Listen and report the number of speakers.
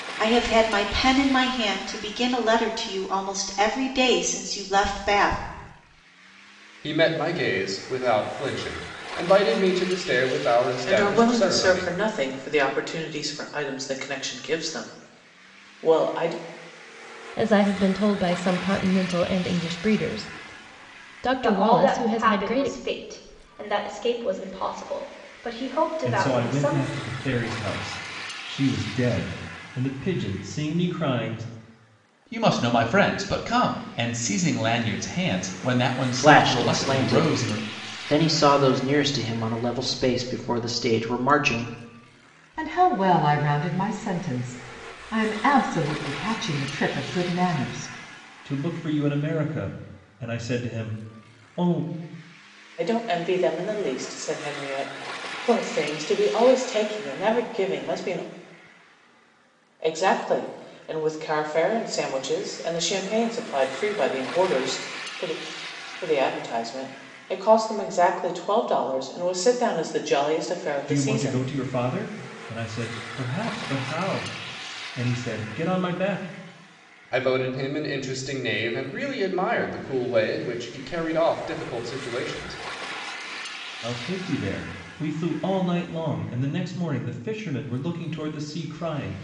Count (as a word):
nine